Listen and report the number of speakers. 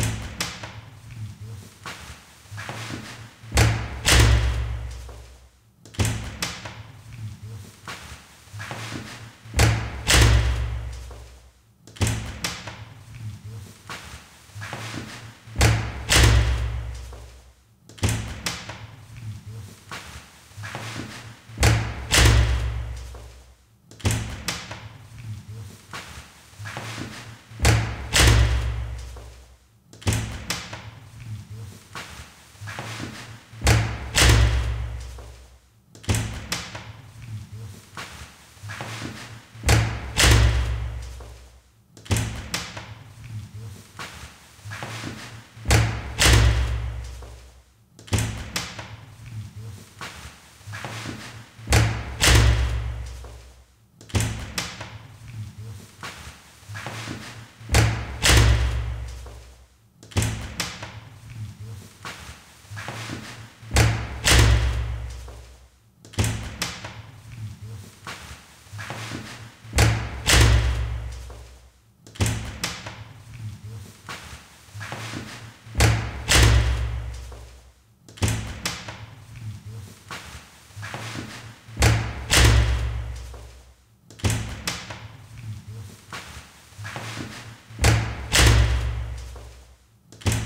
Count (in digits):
0